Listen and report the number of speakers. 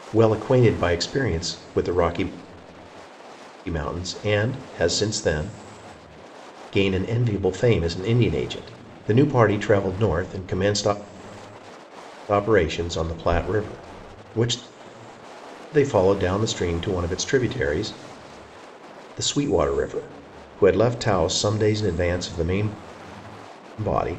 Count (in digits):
1